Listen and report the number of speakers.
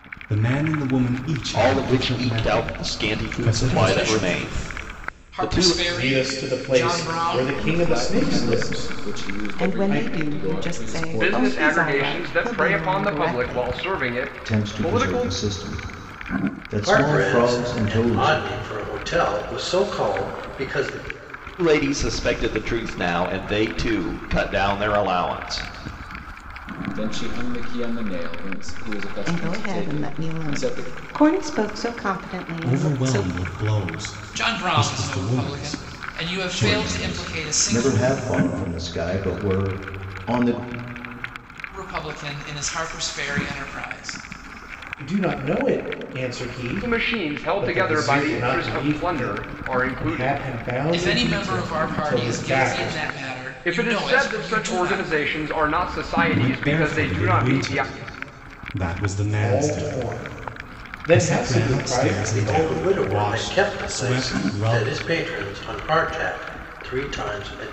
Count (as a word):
nine